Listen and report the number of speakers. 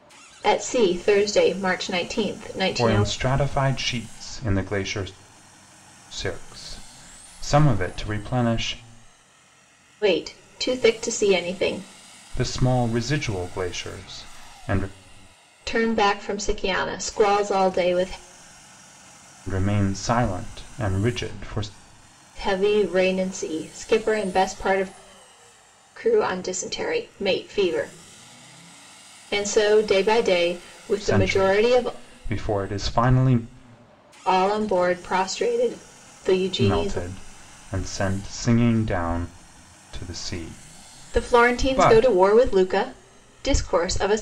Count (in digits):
2